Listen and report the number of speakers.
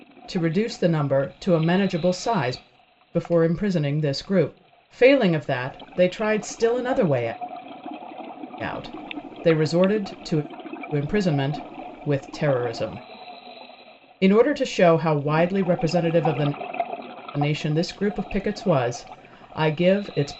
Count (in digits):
1